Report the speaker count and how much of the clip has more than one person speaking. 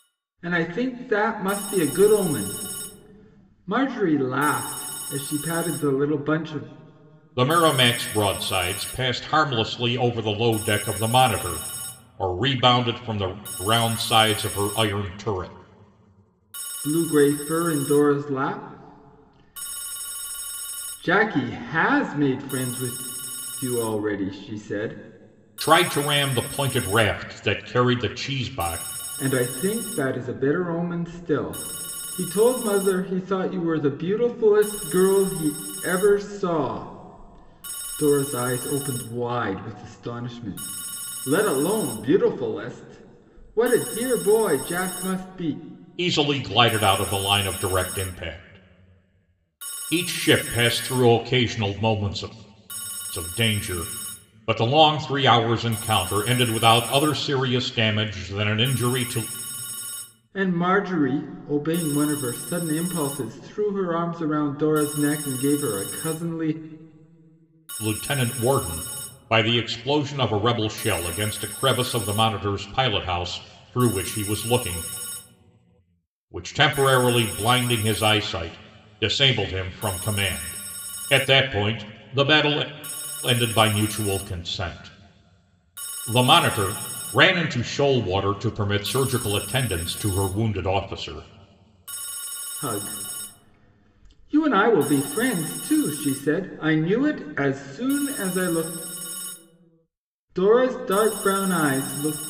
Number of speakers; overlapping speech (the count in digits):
2, no overlap